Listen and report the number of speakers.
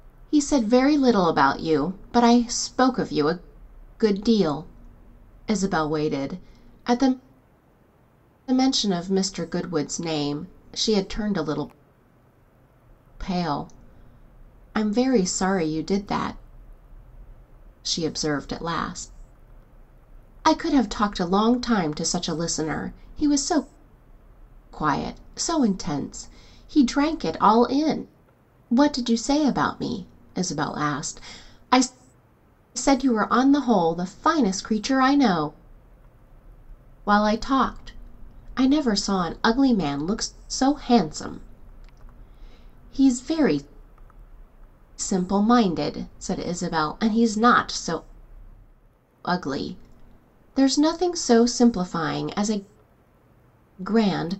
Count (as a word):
one